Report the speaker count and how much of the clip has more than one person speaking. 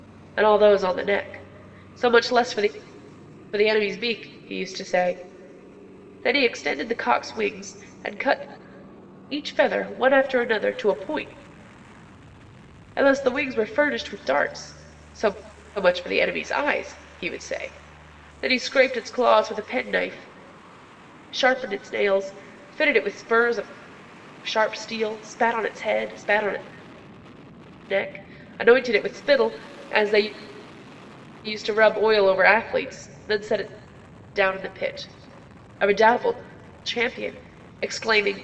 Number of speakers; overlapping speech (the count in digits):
1, no overlap